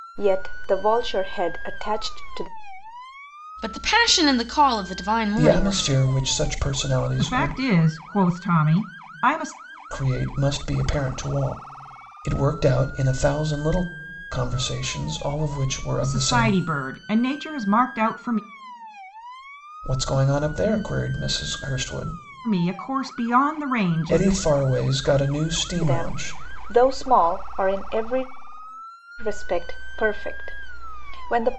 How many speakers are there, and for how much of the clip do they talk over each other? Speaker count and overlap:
four, about 8%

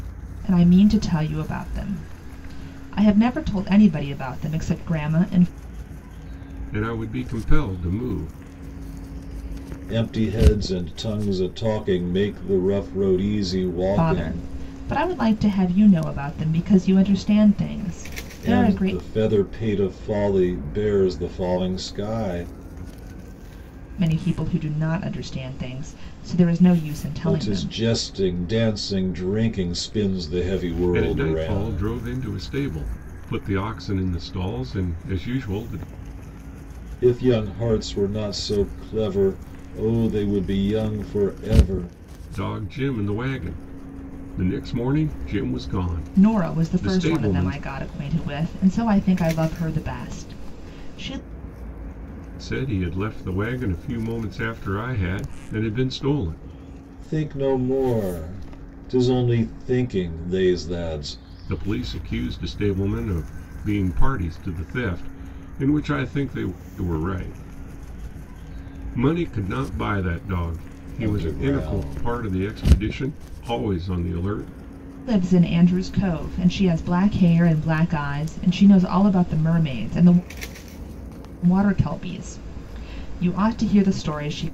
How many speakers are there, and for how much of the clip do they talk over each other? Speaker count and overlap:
three, about 7%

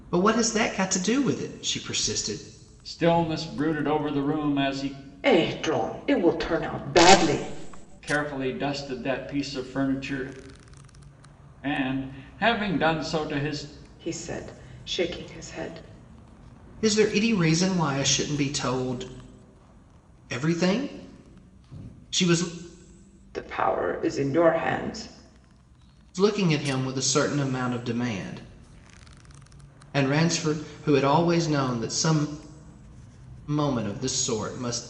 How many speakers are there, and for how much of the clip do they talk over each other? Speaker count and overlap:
three, no overlap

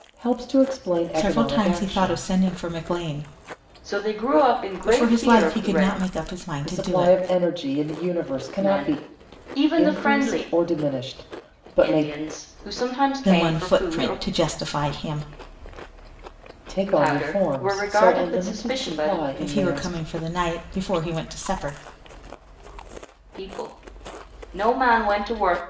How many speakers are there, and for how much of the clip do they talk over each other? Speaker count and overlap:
three, about 33%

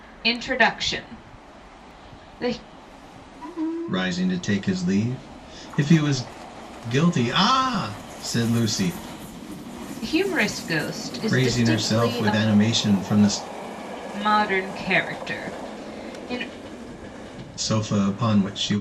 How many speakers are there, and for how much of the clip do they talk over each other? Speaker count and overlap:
two, about 6%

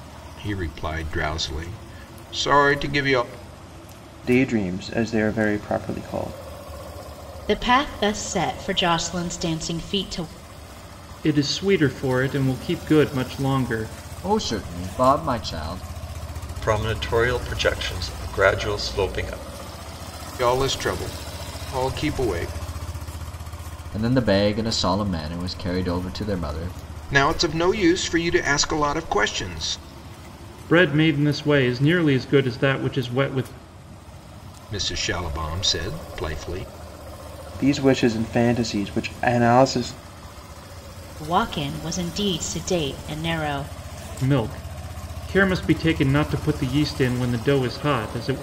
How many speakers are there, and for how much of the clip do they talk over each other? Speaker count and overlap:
six, no overlap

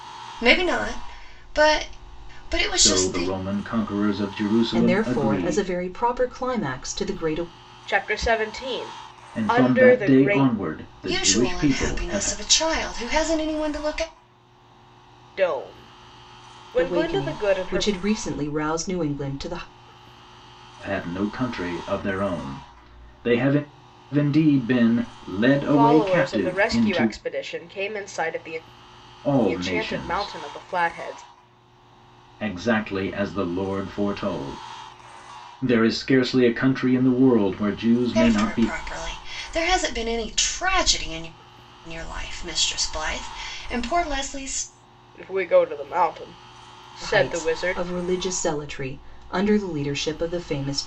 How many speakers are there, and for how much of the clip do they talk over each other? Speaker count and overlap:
four, about 18%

